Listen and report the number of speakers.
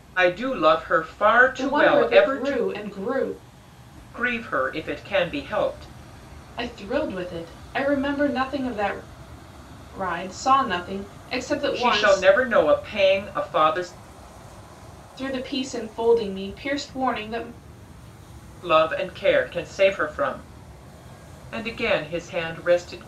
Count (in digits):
2